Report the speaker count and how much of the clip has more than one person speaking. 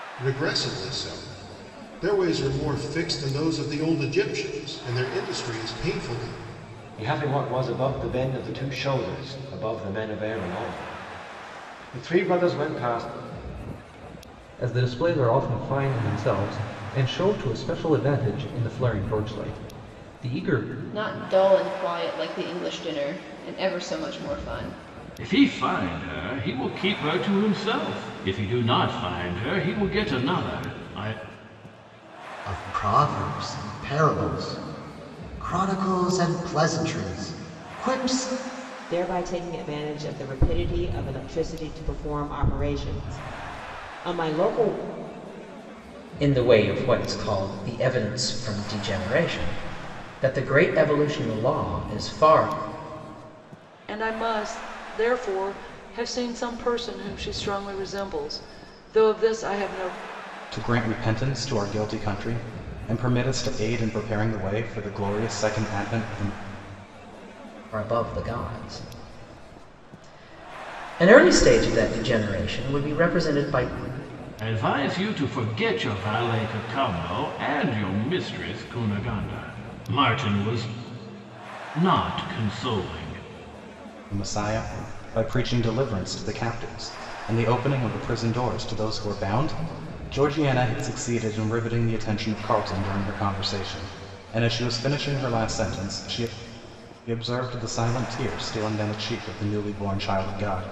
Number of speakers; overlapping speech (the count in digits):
10, no overlap